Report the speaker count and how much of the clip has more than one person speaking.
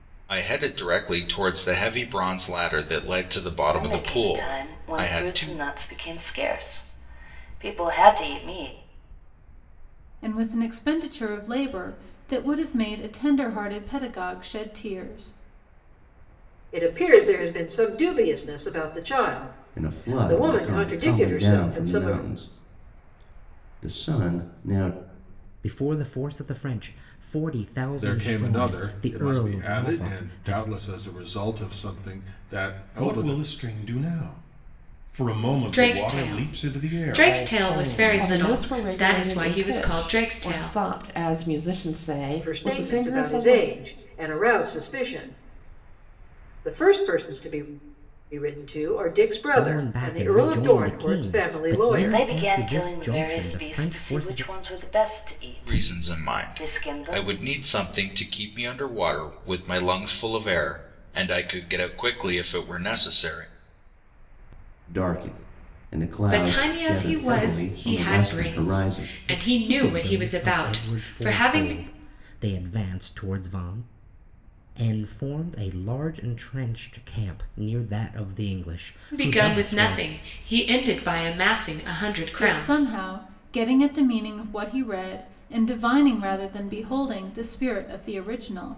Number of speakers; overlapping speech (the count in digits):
10, about 31%